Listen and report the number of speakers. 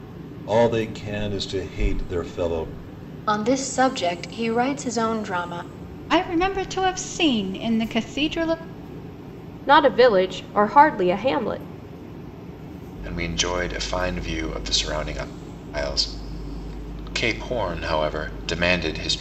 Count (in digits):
5